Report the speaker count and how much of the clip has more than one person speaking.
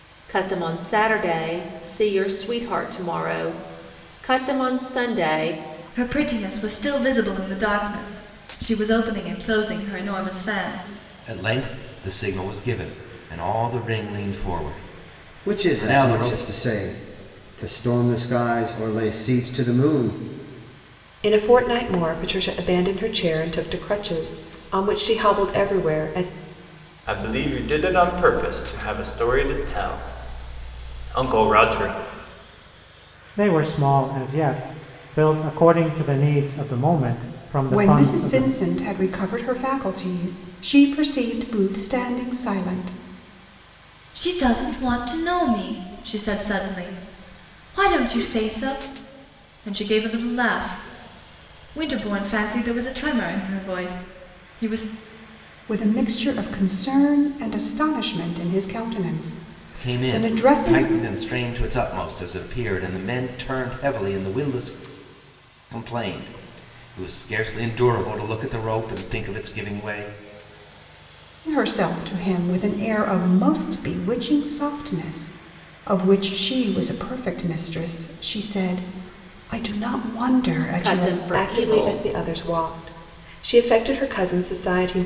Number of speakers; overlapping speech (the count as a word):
eight, about 5%